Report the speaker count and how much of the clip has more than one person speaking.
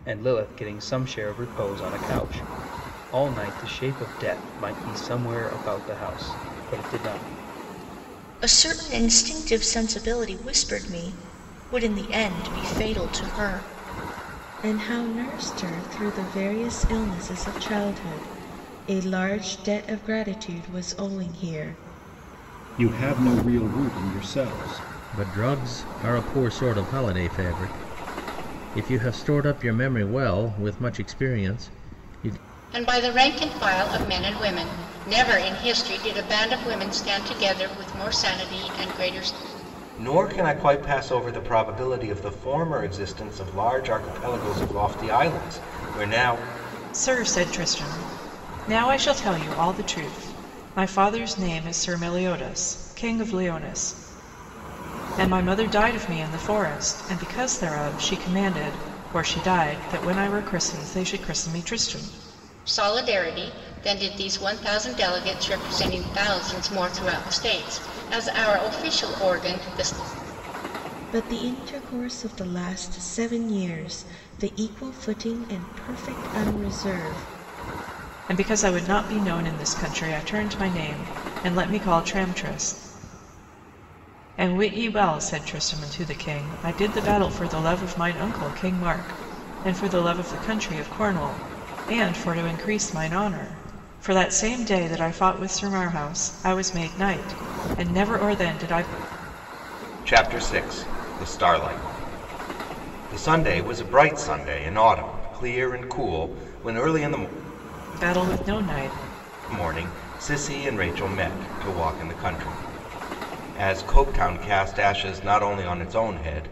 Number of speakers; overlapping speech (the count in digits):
8, no overlap